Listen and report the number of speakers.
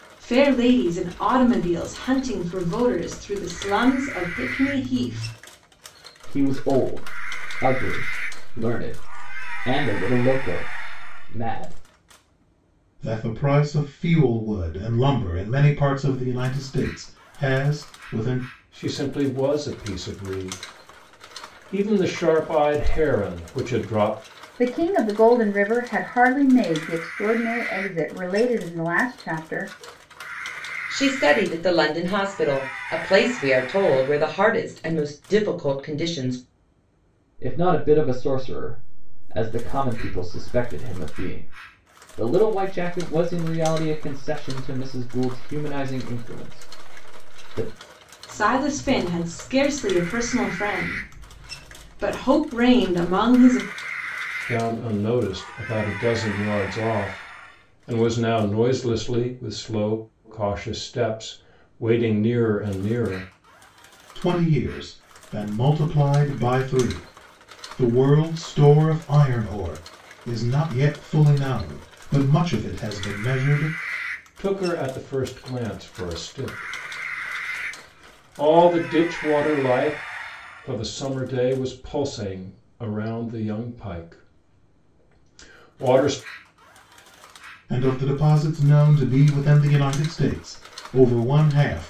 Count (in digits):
6